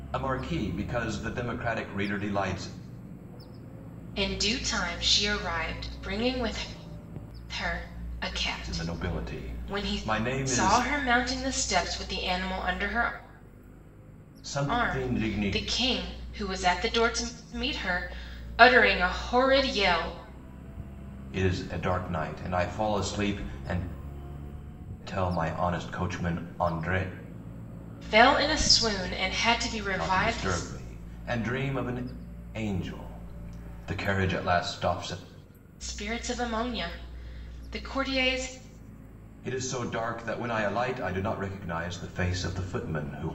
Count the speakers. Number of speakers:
two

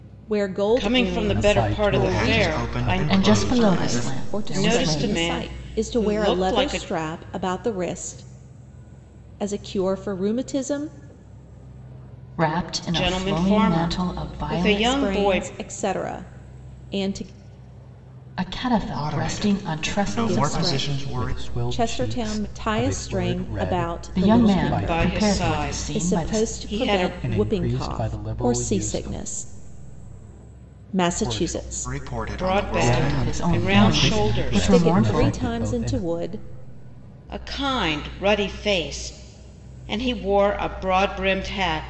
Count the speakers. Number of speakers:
five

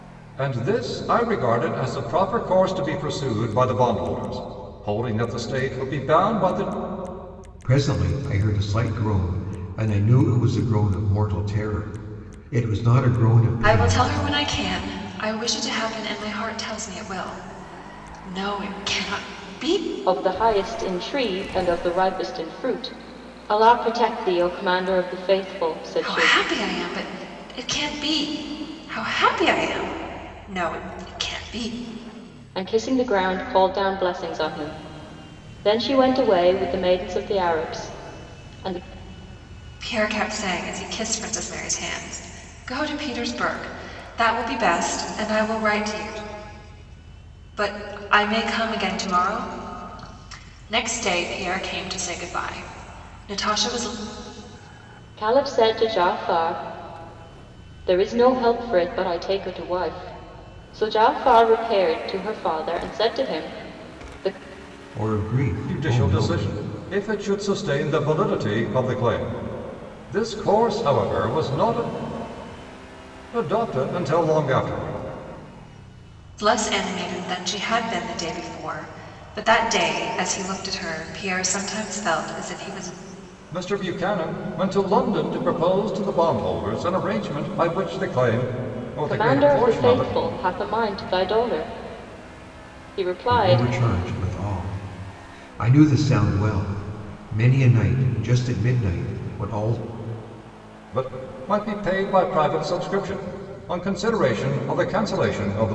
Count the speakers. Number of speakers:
four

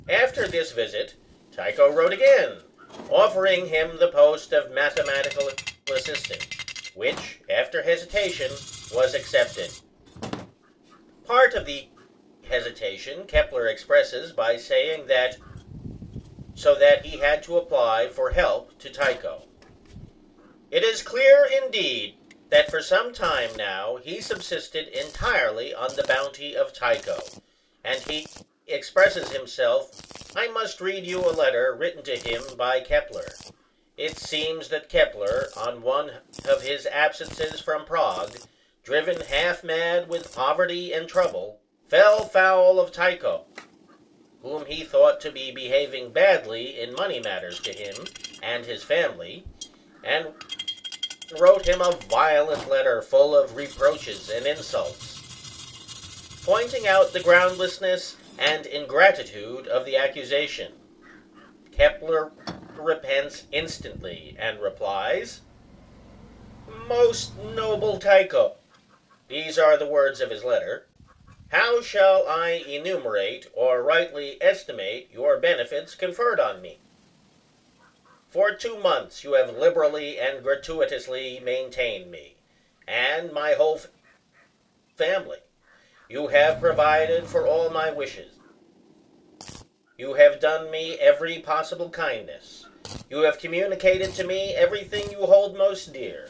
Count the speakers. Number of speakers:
one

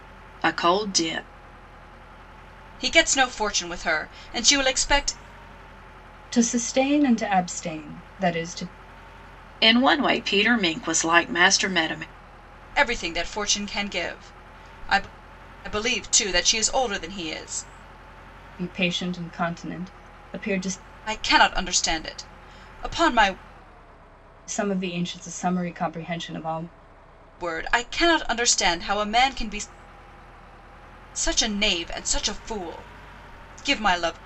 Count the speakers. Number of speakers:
three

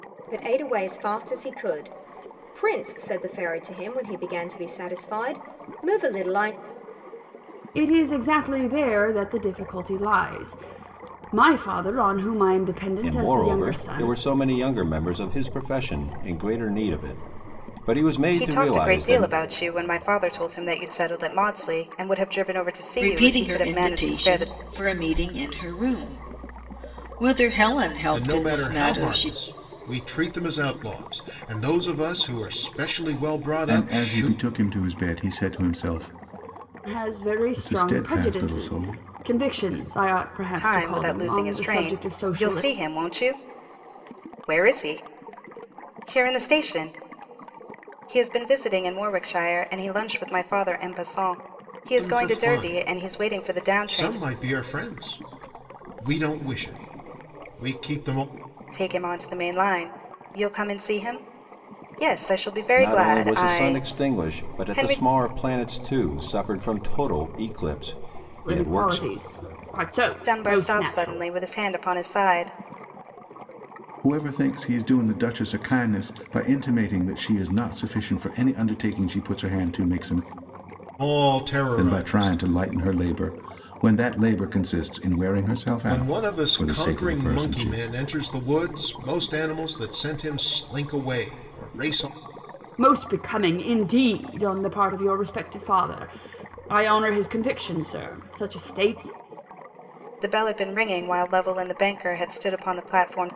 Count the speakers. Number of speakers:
seven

